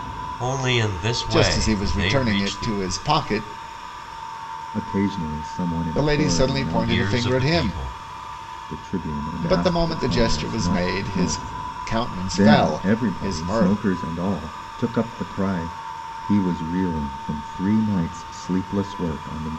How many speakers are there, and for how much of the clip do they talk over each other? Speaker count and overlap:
3, about 39%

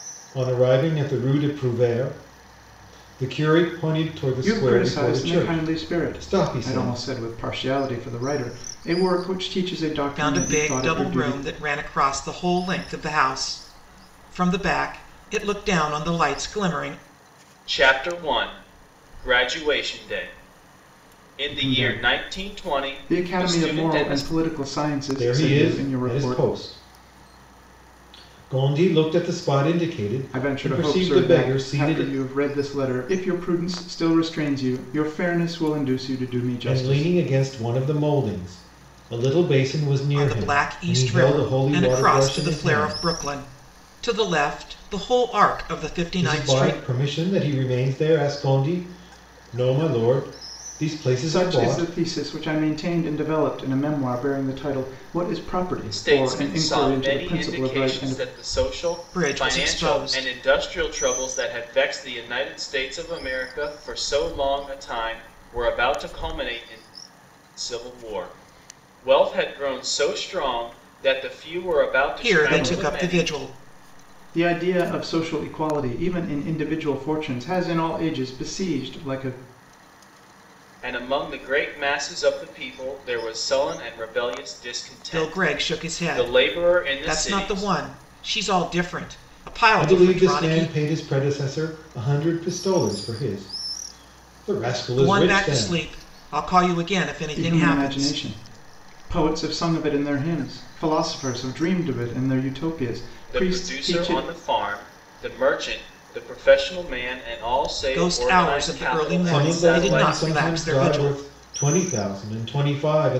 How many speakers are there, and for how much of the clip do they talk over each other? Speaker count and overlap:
4, about 26%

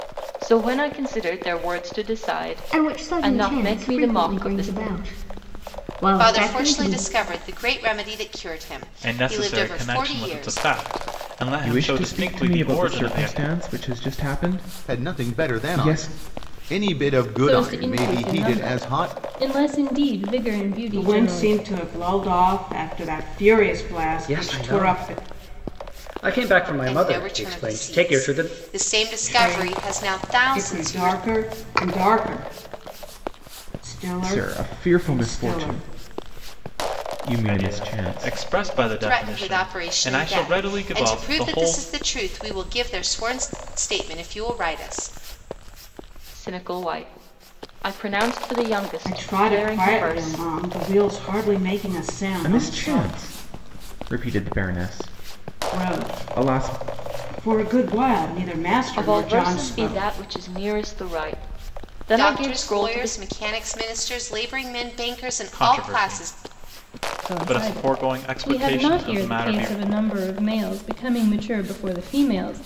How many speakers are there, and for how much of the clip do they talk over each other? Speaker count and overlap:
9, about 41%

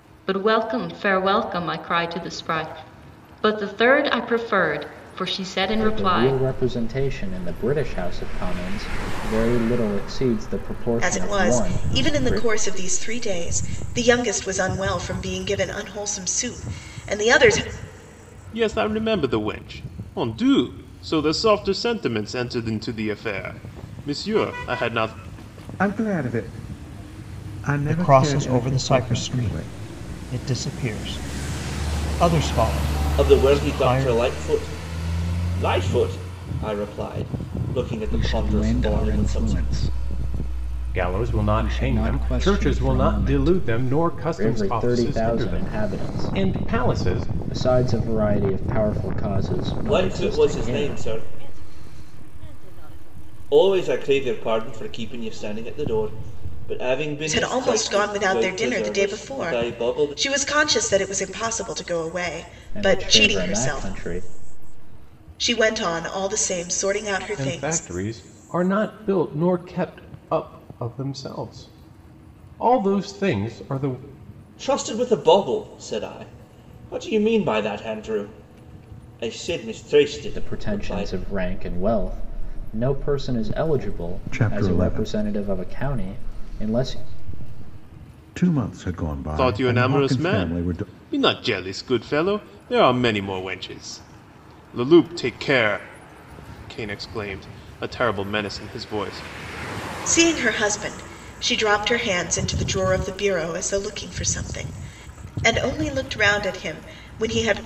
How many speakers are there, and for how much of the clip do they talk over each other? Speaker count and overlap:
10, about 26%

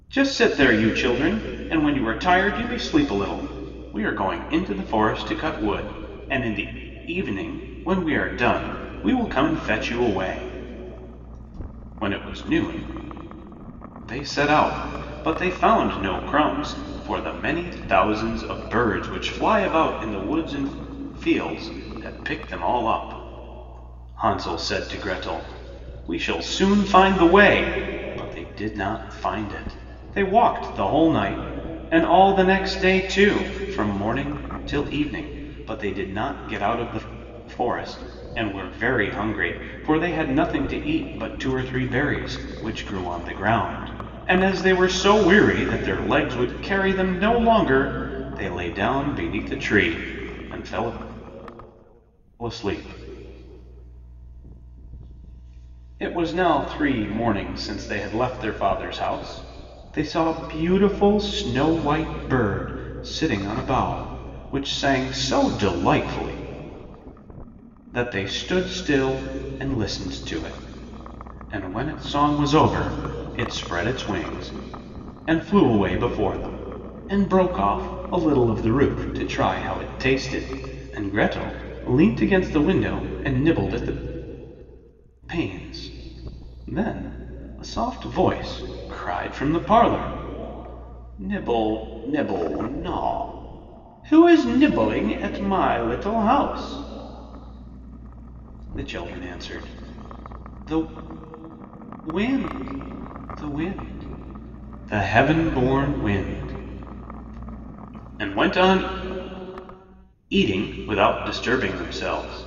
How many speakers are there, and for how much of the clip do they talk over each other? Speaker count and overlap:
1, no overlap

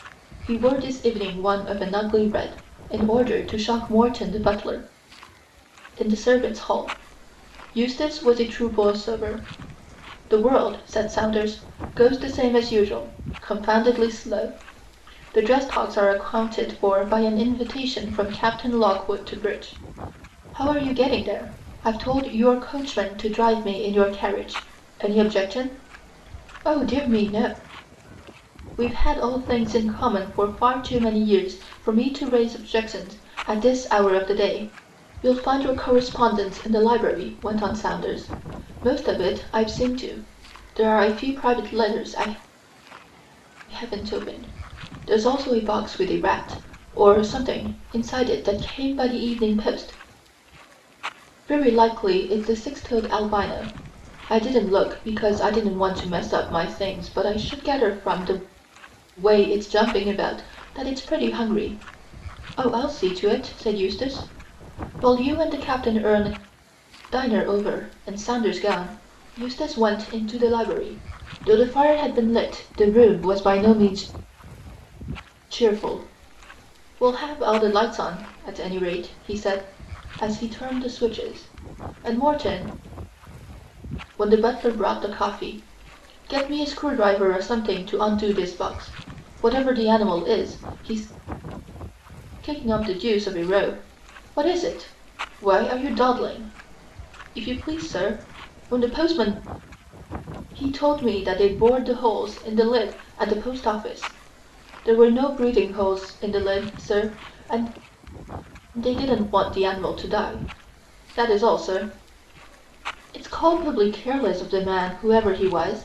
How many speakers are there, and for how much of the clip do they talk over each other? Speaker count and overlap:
1, no overlap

